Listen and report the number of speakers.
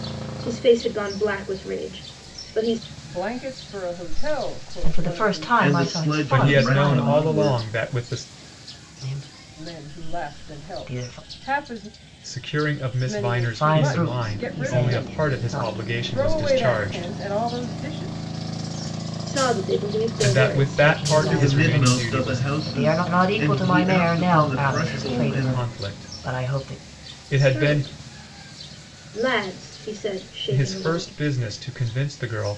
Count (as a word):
five